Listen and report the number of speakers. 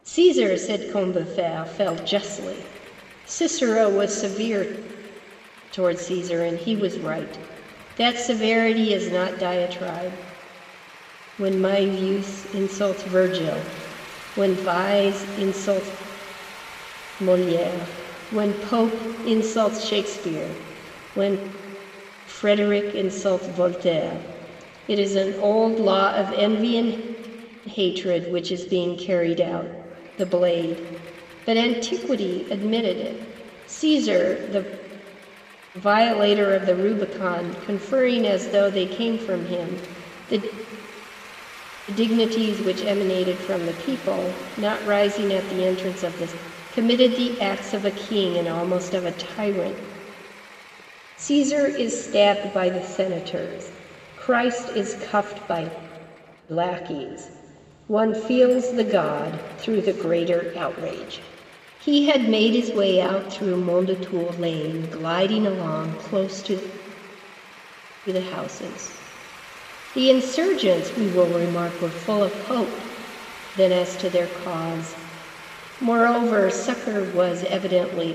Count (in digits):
1